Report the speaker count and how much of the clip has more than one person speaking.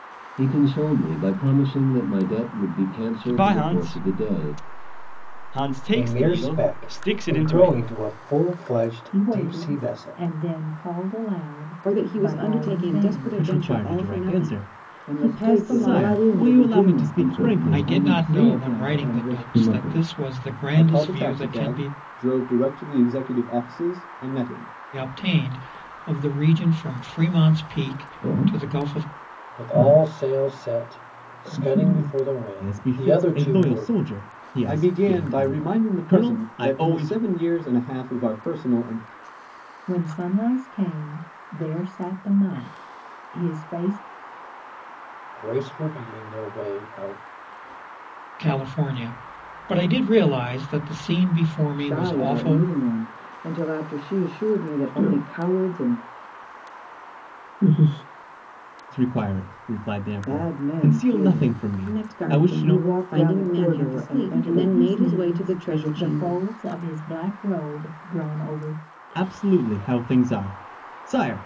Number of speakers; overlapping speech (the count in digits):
10, about 42%